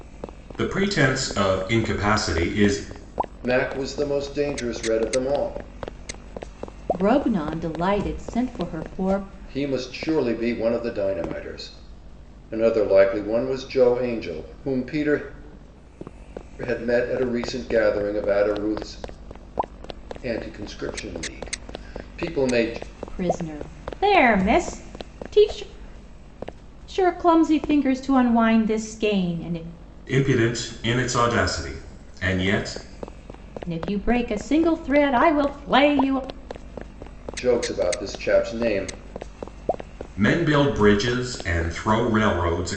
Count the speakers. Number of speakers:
3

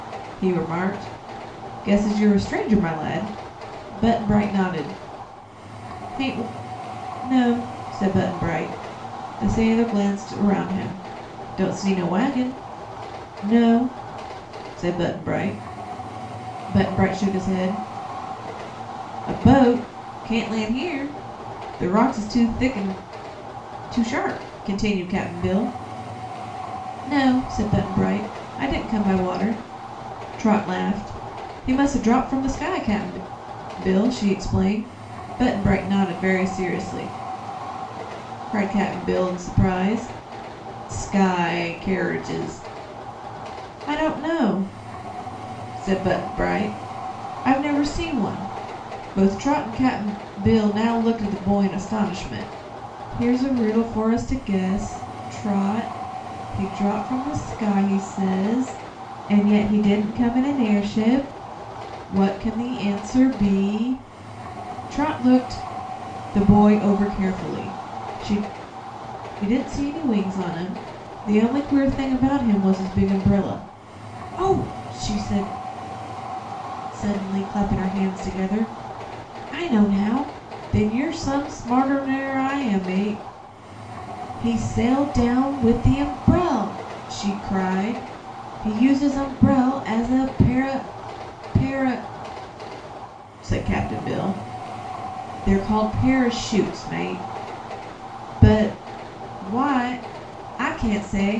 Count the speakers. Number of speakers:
1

